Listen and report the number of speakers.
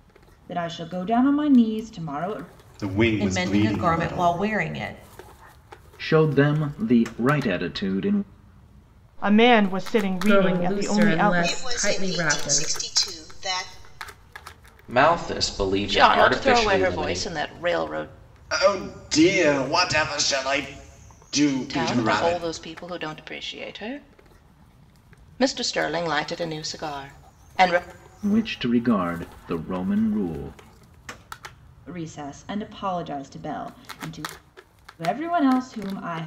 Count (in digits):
9